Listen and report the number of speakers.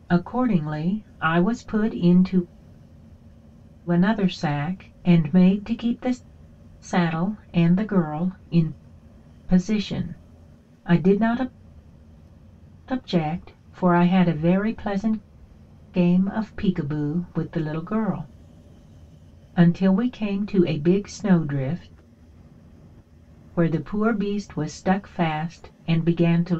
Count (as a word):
one